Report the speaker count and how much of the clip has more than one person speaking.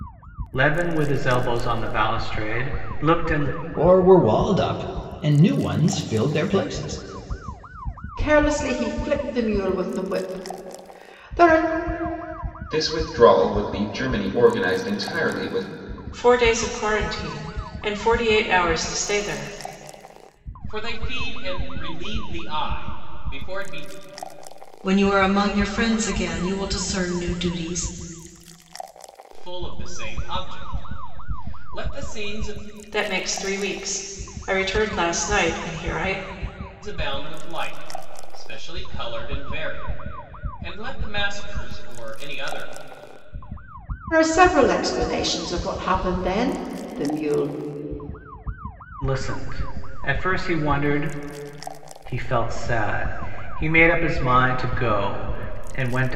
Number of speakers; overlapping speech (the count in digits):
7, no overlap